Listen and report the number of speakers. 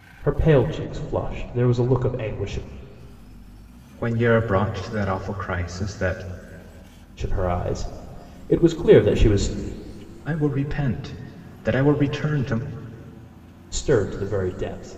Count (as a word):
two